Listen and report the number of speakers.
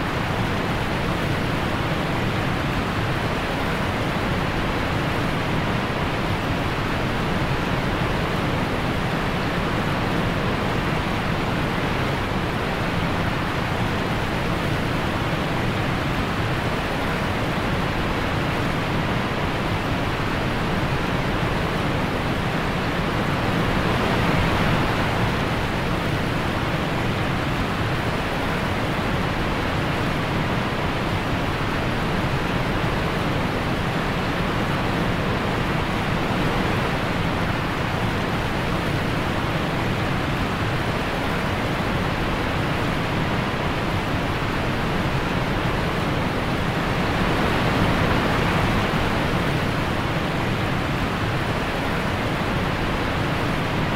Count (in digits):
0